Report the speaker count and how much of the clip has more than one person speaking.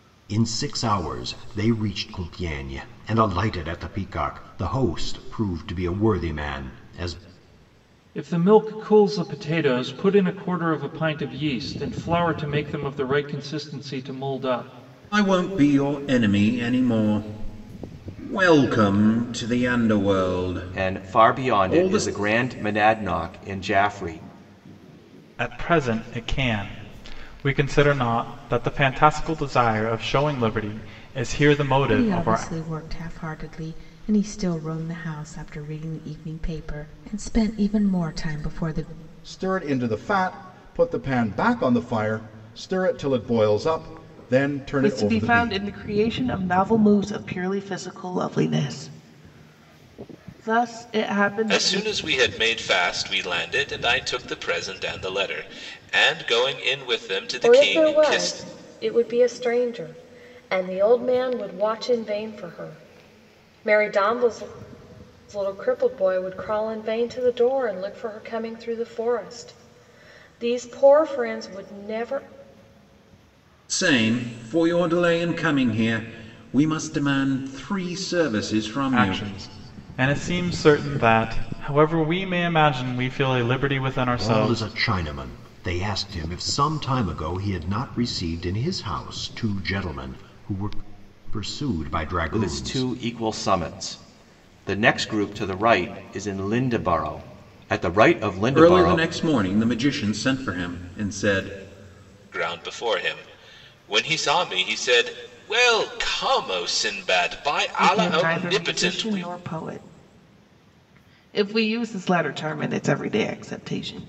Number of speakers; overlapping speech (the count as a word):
ten, about 7%